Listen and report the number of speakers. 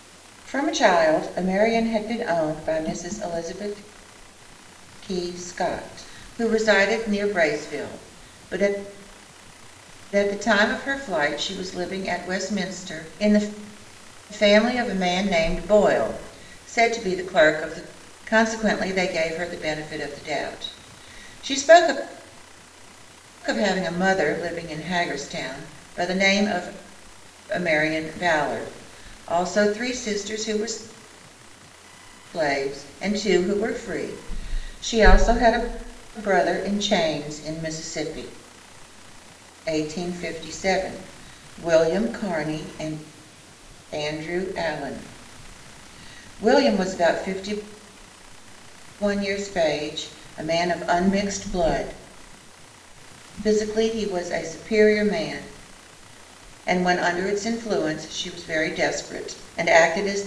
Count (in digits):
1